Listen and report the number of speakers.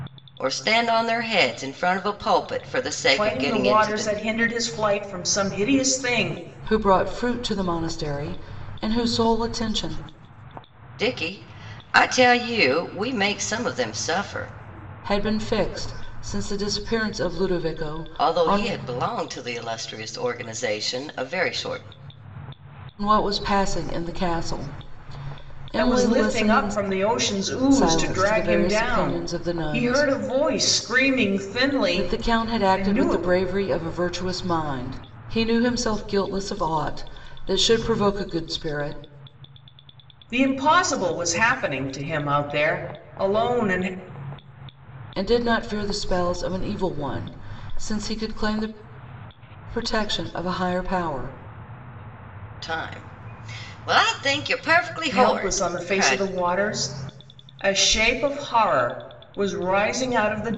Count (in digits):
3